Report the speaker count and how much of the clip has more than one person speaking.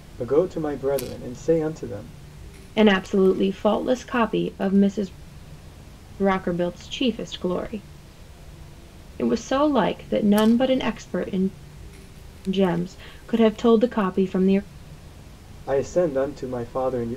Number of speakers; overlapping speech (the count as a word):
two, no overlap